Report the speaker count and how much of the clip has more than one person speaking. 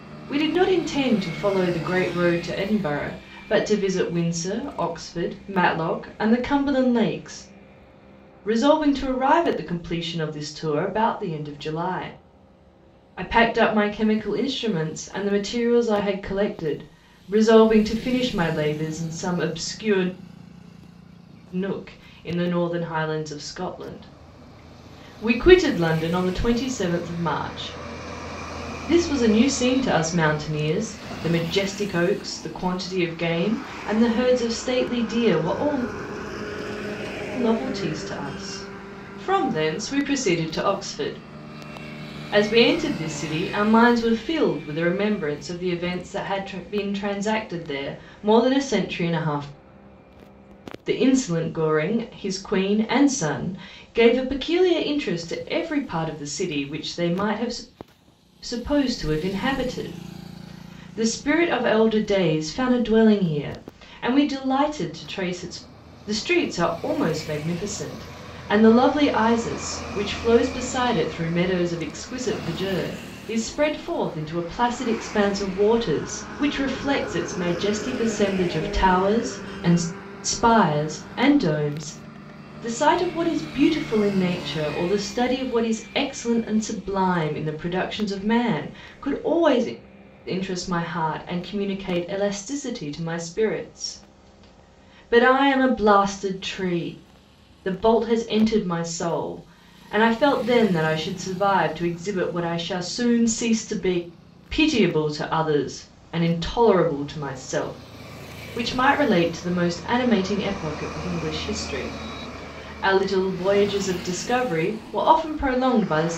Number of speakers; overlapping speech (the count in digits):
1, no overlap